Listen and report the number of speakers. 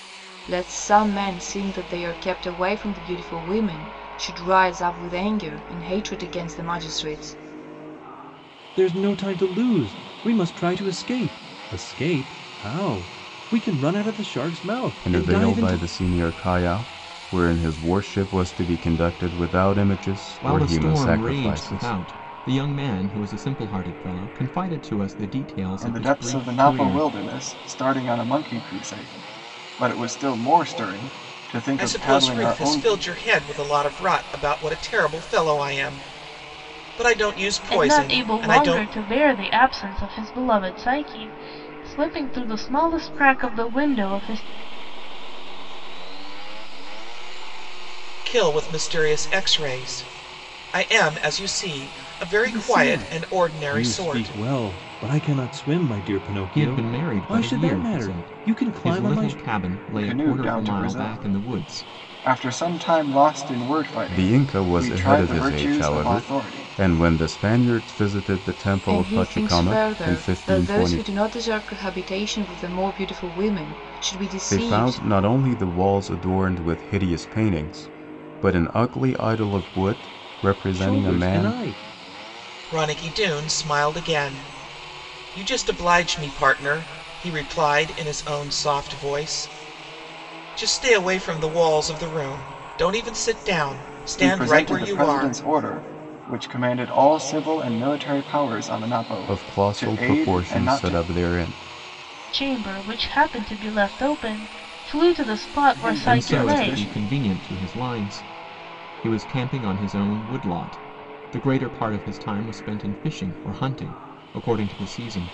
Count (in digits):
8